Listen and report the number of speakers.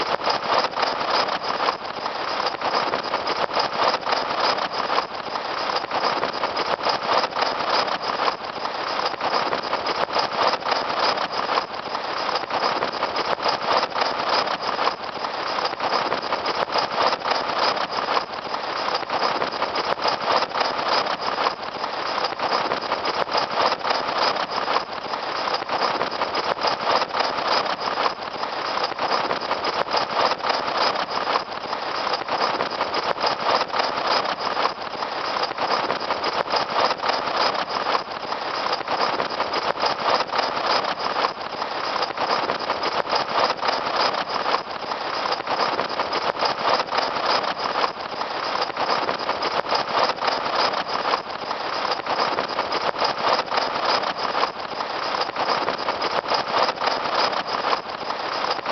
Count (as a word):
zero